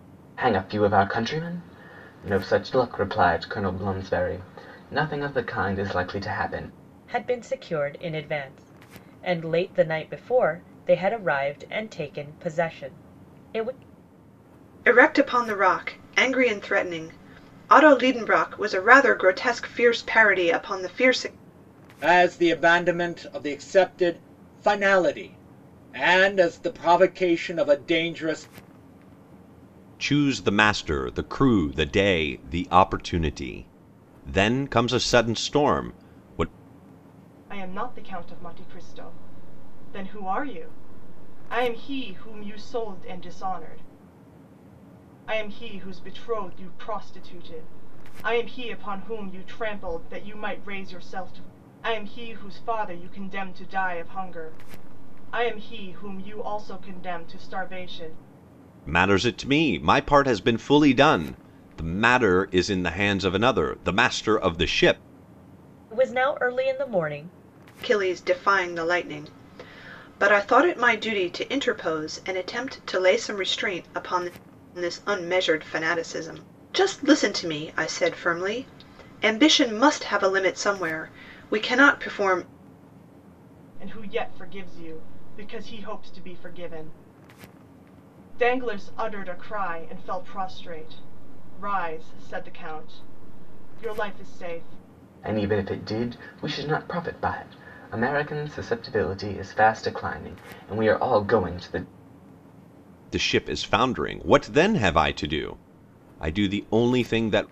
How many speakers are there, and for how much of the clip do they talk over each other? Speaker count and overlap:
six, no overlap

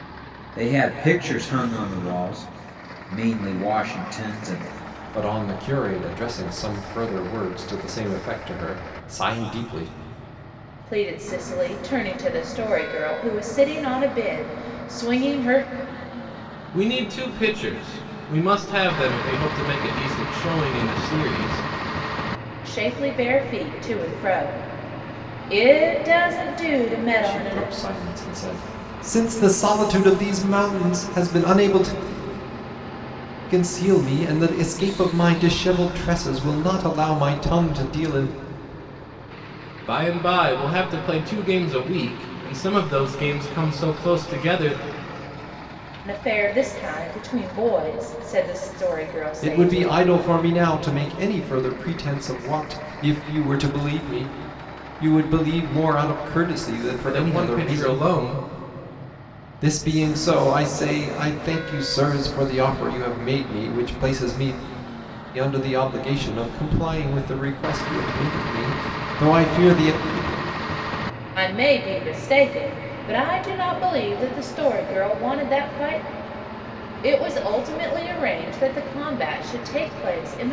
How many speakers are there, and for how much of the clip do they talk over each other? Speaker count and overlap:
four, about 3%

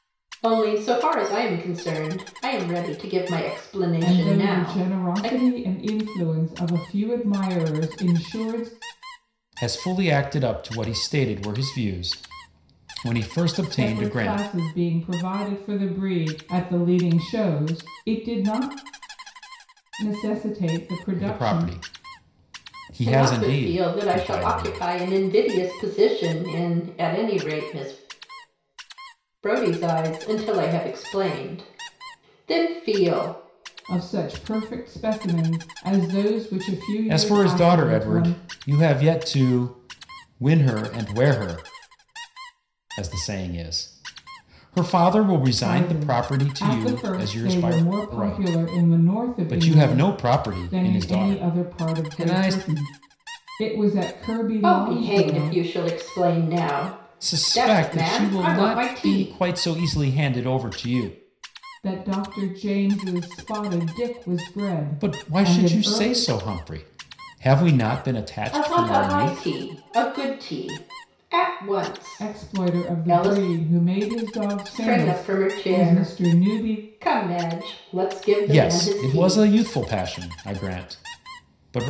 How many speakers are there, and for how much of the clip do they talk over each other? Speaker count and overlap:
three, about 27%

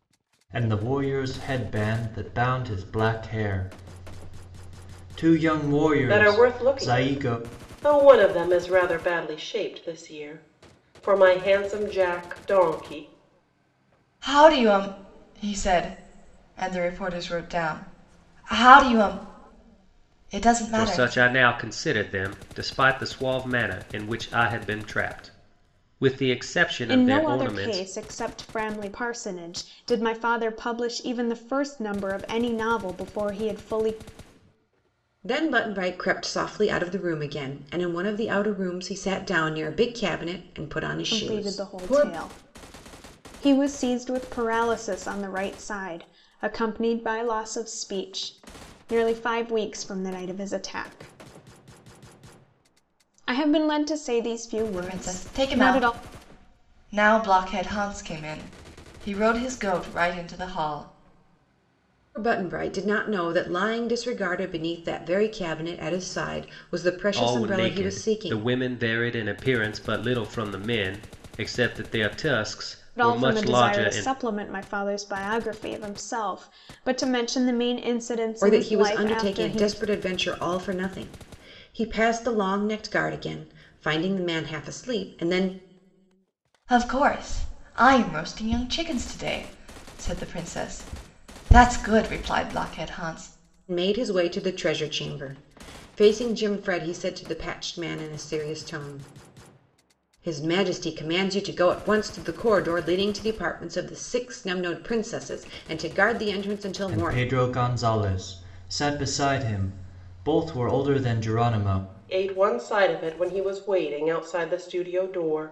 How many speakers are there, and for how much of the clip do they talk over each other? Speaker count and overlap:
six, about 9%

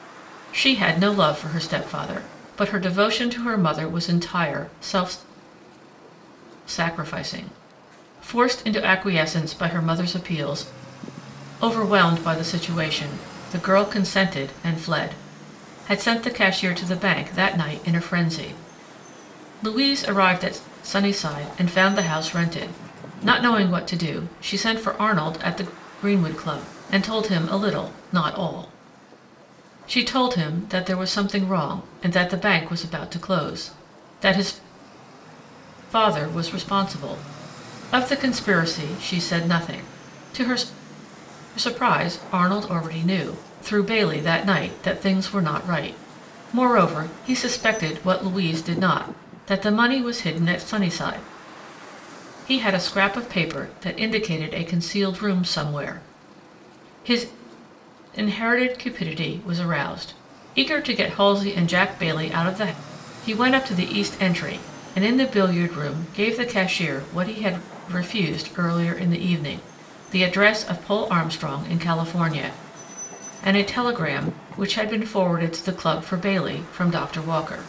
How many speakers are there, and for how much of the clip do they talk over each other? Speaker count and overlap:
one, no overlap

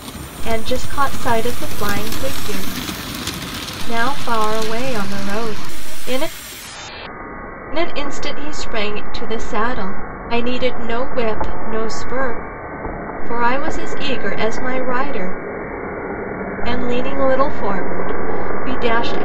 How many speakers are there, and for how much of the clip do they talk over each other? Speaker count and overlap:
one, no overlap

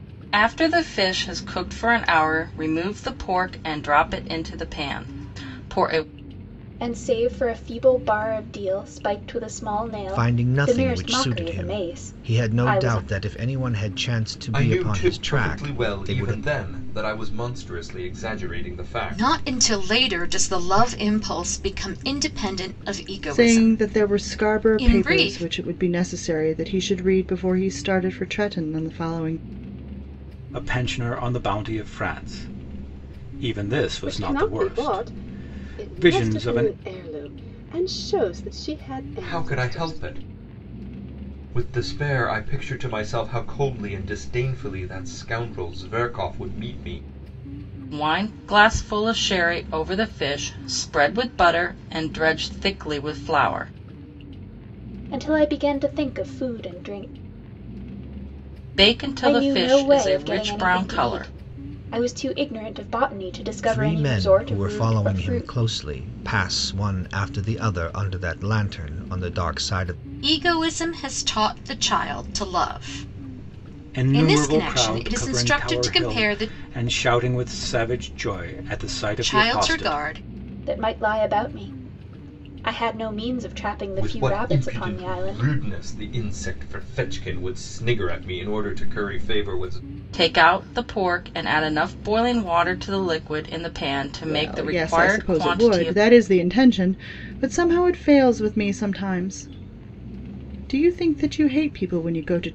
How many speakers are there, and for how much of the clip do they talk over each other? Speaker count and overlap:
eight, about 23%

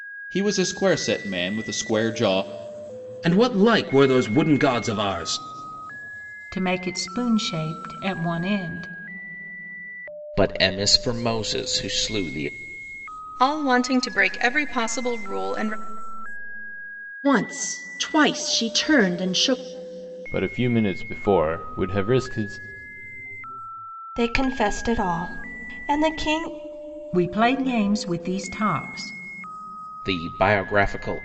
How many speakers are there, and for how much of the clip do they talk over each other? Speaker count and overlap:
eight, no overlap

